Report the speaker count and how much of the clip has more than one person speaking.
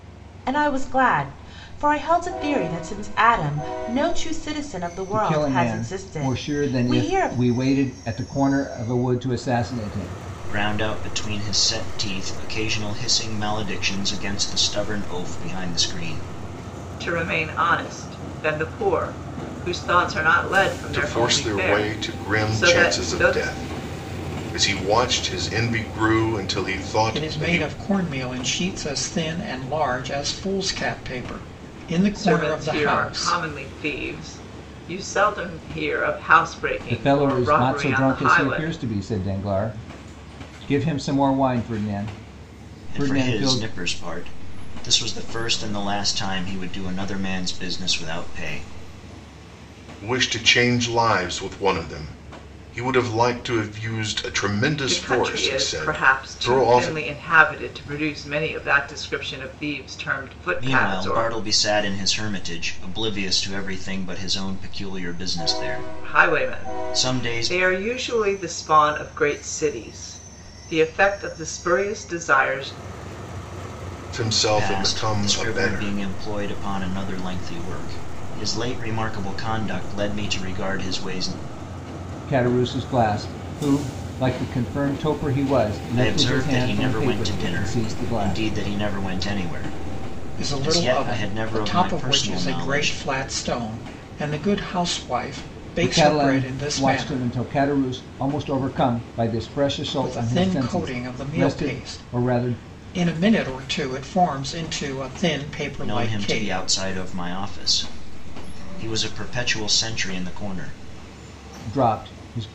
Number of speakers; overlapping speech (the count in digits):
6, about 23%